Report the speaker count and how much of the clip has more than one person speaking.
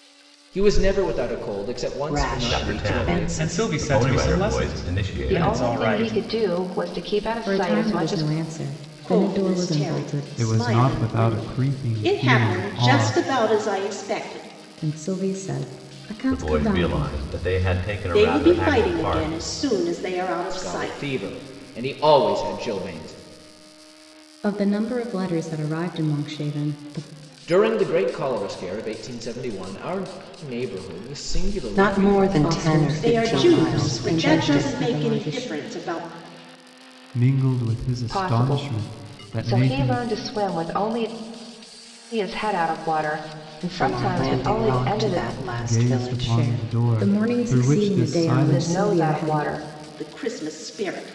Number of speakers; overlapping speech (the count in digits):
8, about 45%